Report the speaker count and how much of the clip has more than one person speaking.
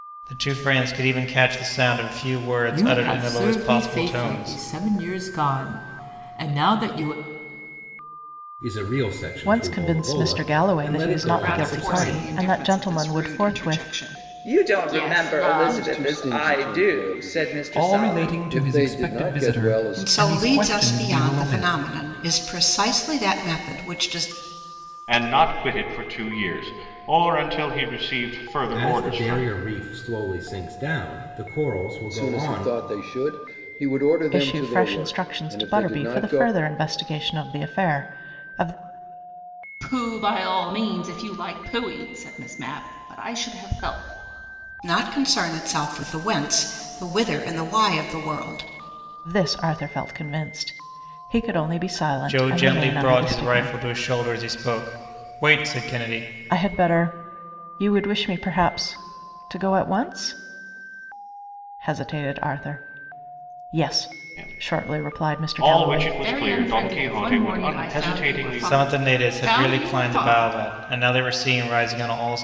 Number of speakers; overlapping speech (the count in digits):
10, about 35%